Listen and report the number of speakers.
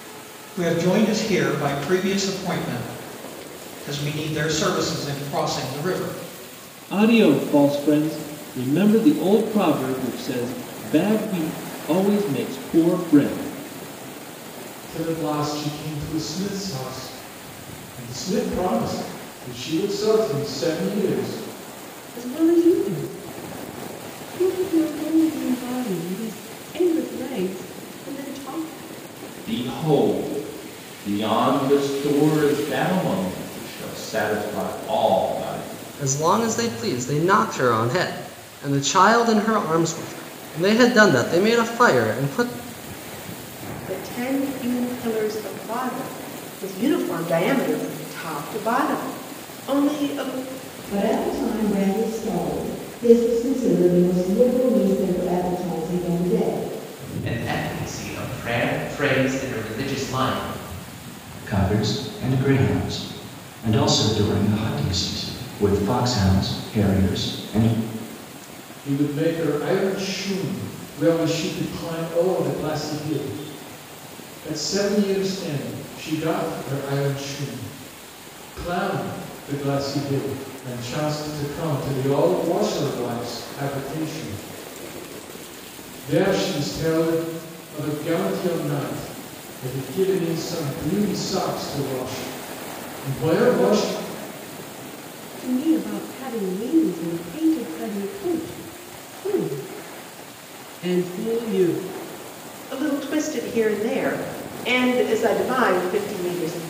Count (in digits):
10